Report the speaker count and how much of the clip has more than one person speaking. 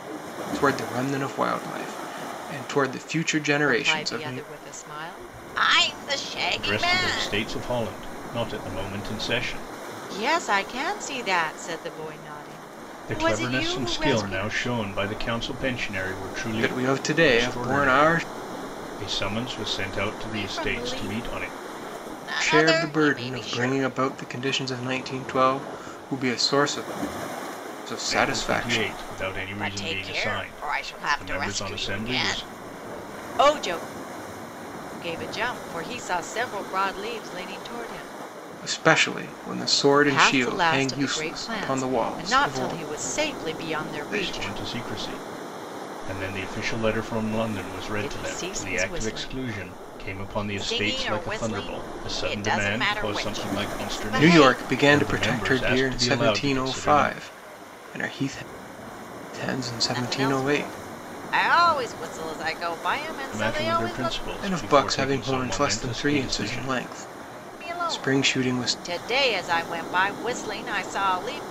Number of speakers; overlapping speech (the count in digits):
3, about 42%